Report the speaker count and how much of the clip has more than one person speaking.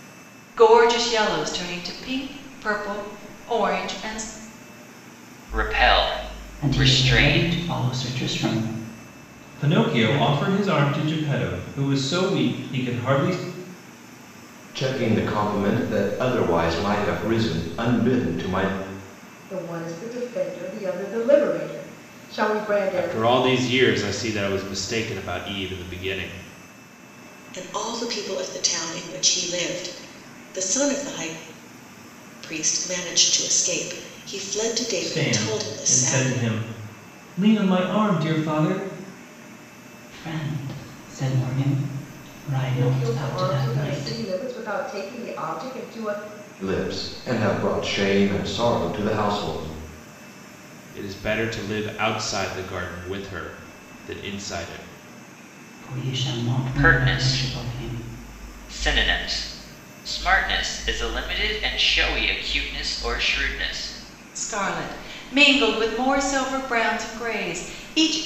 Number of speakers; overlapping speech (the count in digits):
8, about 9%